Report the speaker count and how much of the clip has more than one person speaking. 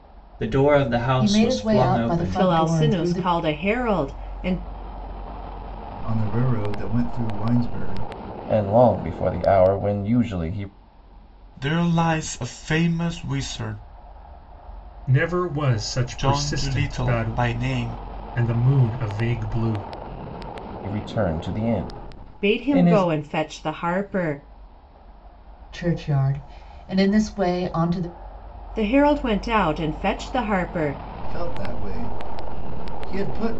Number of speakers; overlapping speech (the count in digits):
7, about 13%